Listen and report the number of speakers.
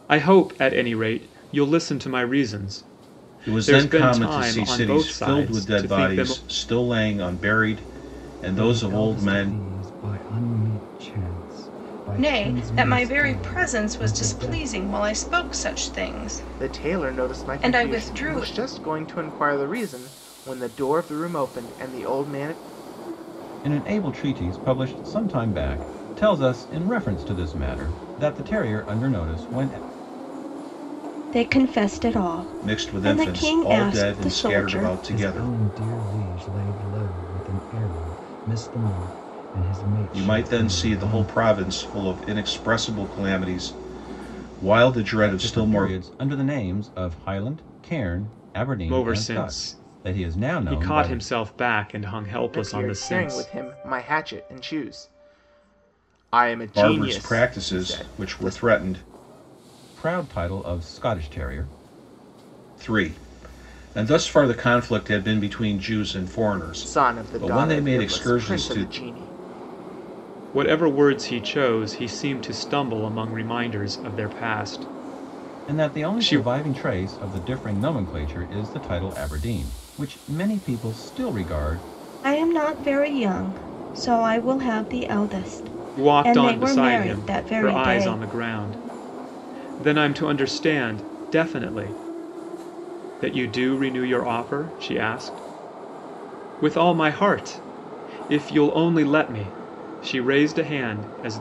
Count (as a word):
seven